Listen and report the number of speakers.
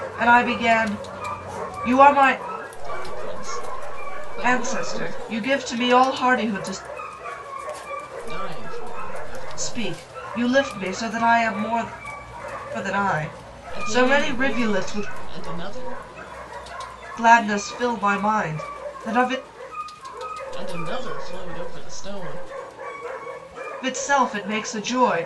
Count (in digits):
2